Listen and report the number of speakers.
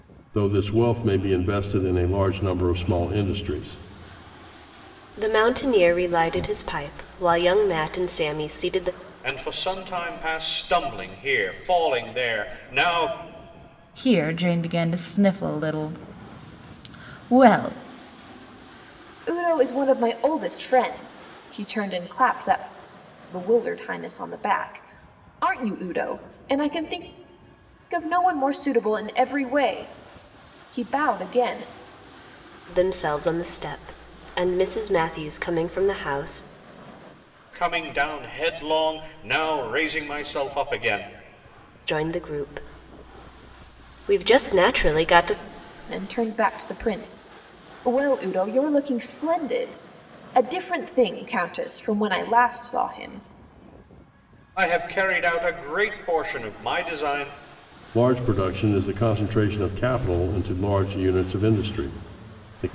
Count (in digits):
5